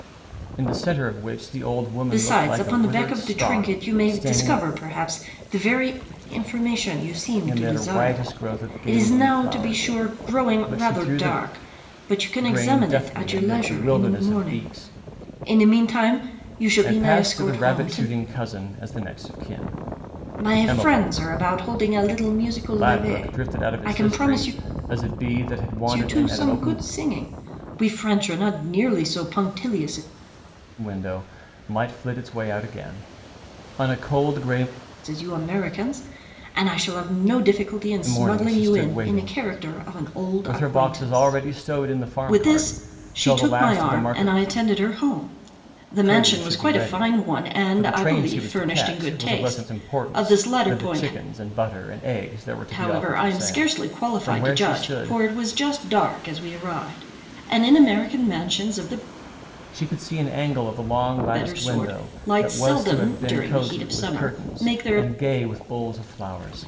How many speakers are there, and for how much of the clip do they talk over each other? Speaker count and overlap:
two, about 44%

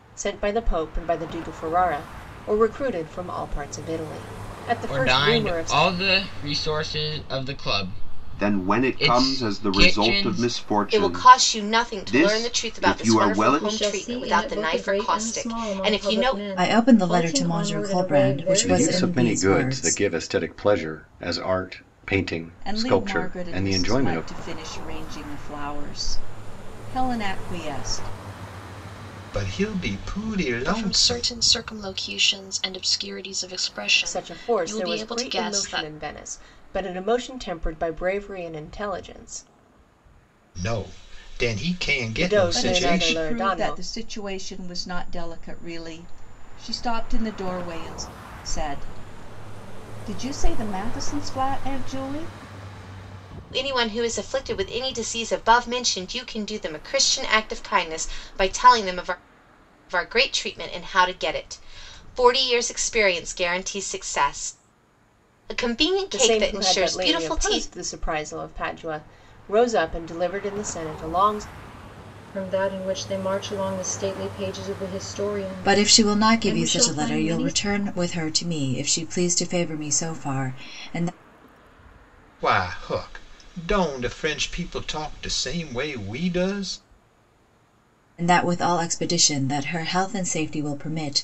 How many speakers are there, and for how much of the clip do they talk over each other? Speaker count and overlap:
ten, about 24%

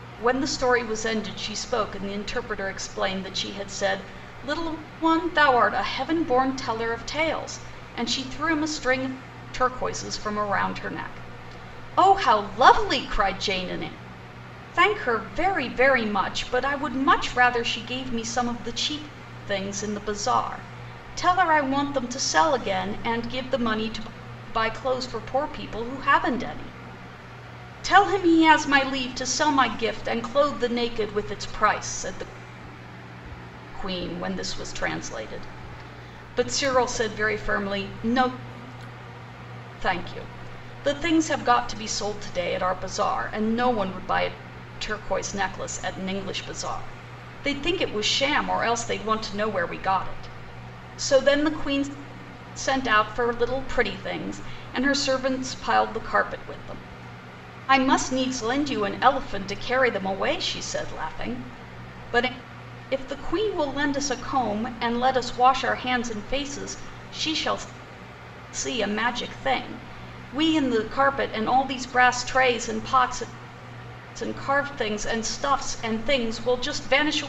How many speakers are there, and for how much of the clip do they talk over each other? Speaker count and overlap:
one, no overlap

